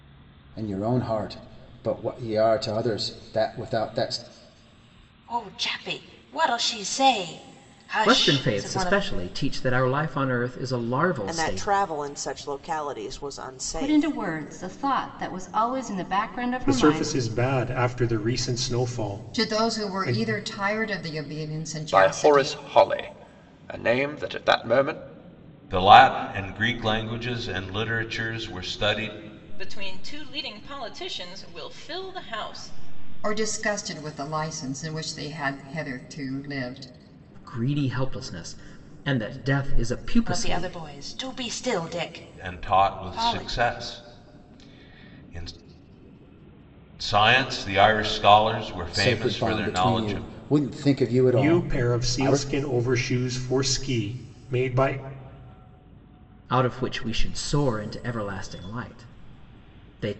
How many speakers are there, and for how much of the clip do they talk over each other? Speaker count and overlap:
10, about 14%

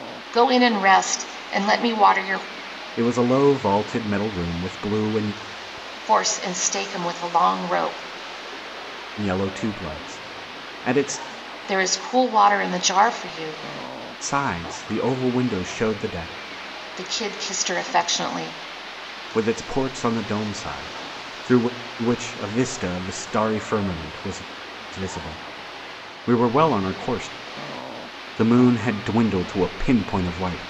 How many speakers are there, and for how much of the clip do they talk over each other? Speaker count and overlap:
2, no overlap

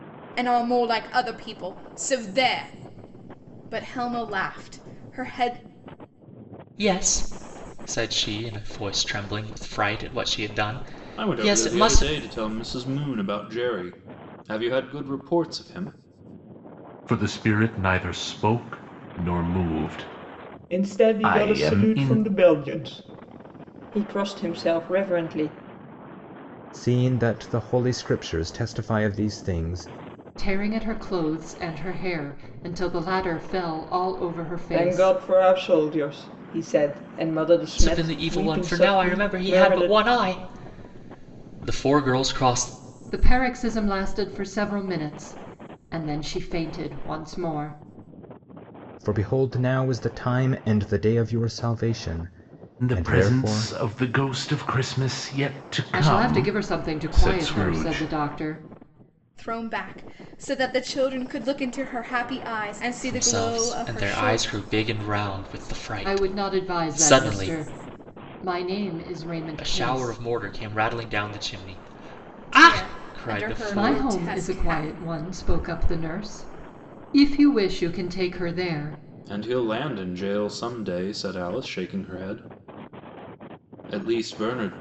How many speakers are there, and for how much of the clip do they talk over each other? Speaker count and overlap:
7, about 17%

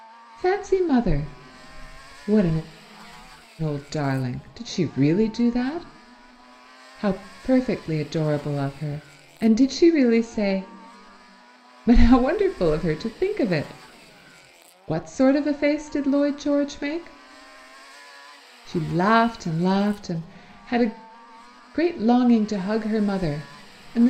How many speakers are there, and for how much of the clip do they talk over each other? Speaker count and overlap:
1, no overlap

